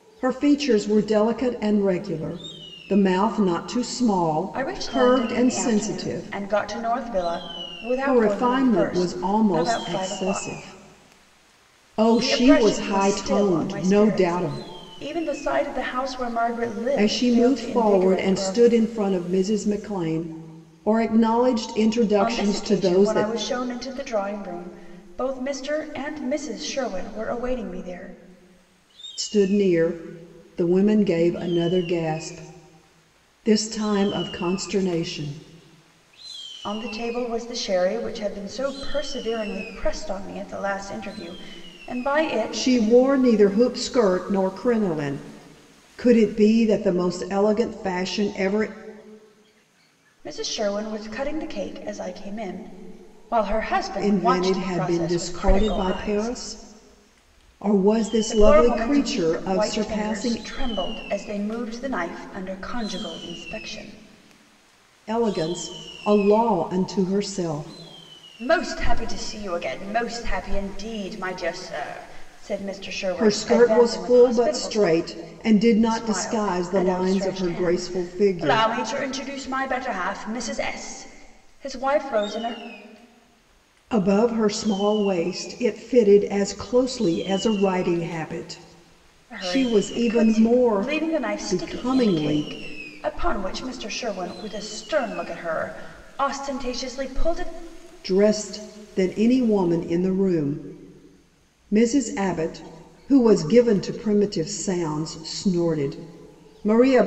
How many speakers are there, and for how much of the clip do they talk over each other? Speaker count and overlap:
2, about 21%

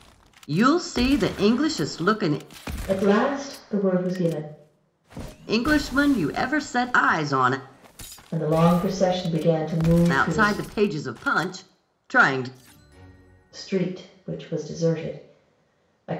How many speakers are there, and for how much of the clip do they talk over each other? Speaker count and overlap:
2, about 3%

